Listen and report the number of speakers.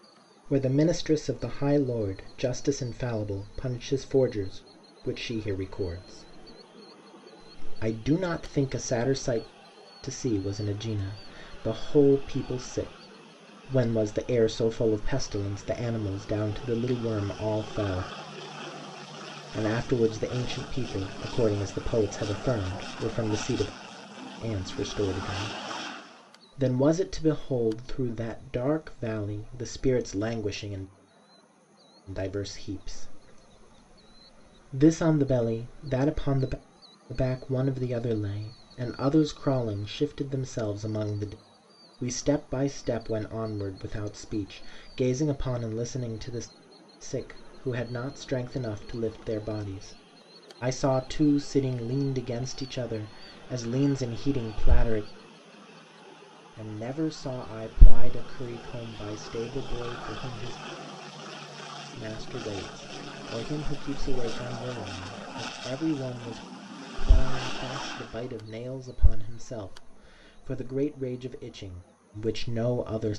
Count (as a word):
one